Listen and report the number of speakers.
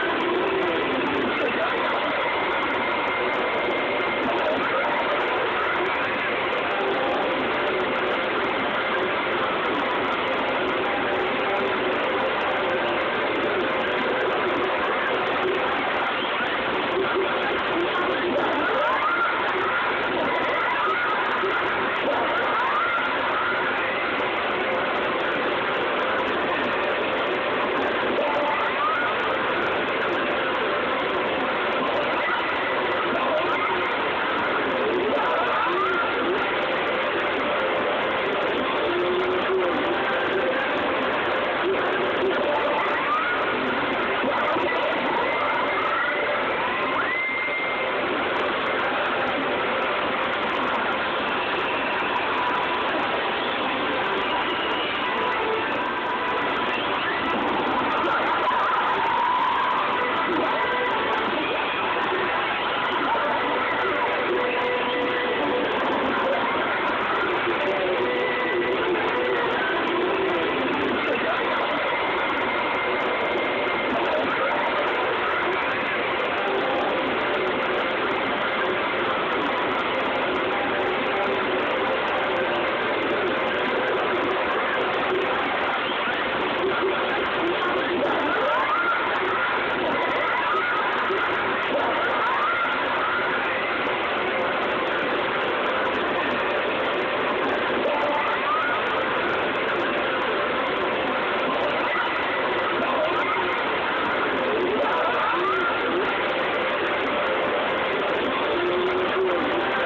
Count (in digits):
0